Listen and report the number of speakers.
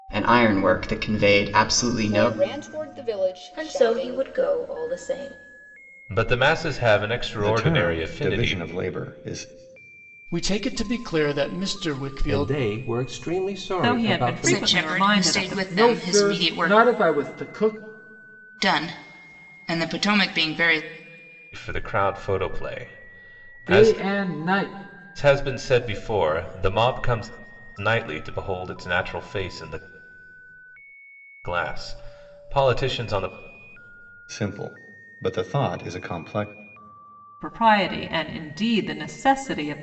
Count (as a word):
ten